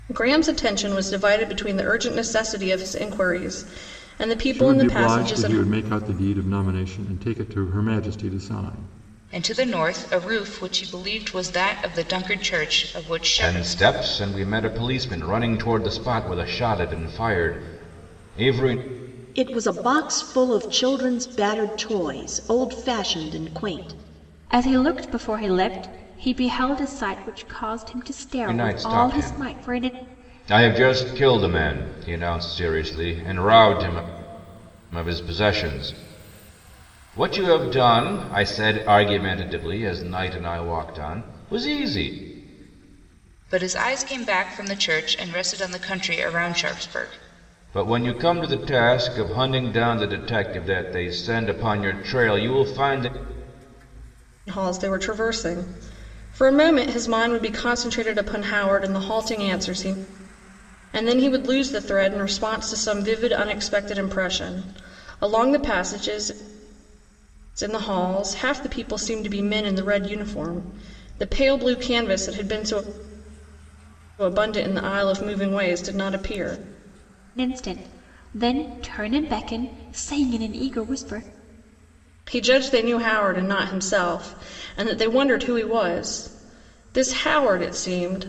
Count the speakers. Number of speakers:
6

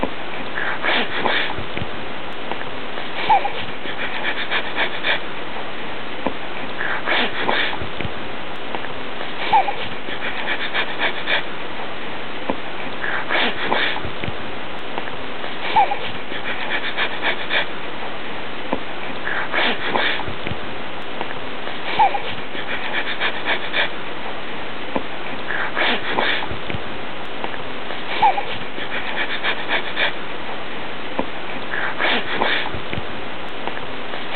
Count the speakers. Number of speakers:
0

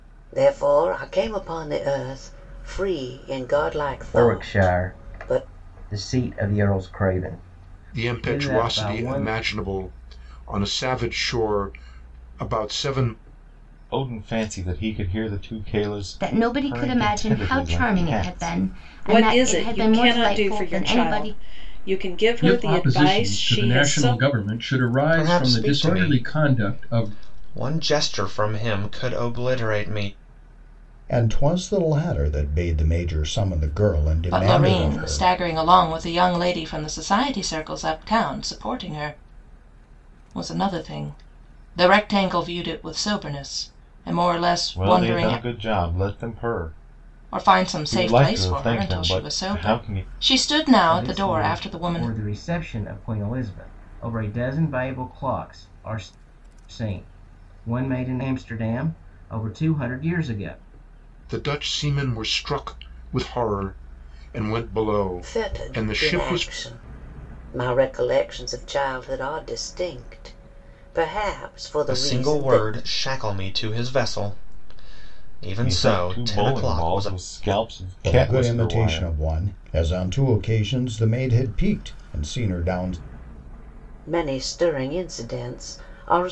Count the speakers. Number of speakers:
10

